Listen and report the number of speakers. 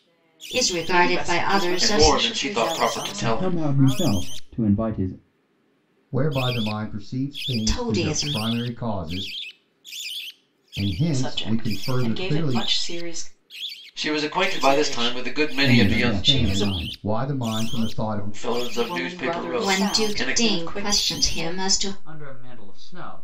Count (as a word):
six